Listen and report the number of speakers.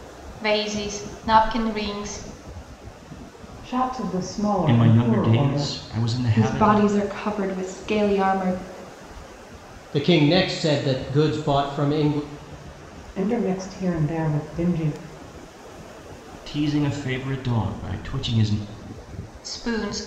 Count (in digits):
5